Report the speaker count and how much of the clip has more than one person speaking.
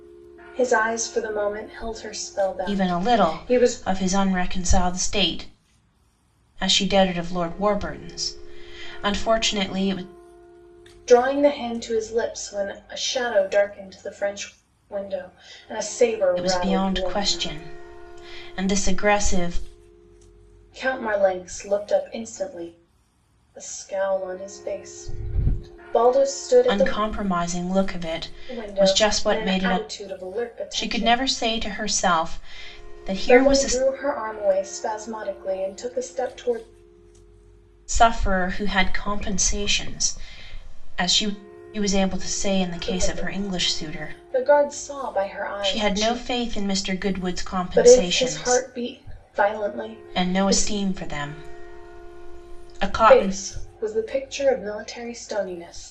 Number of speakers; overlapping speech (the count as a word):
two, about 16%